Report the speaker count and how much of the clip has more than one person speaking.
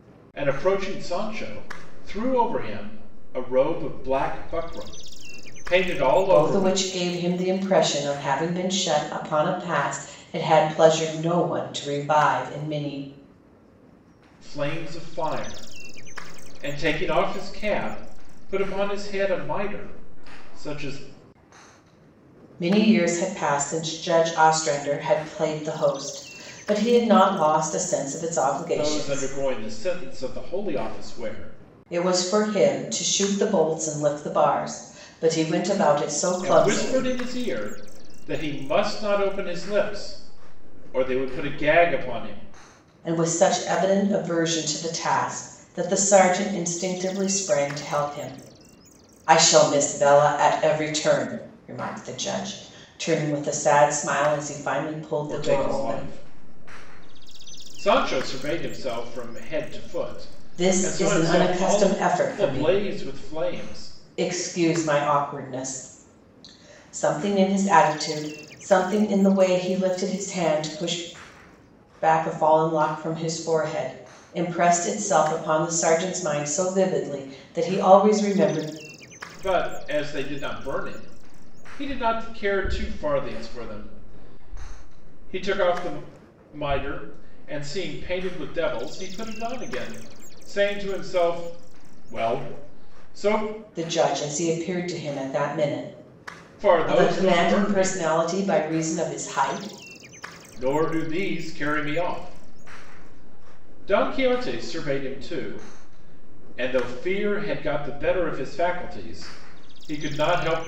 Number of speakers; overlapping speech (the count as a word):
two, about 5%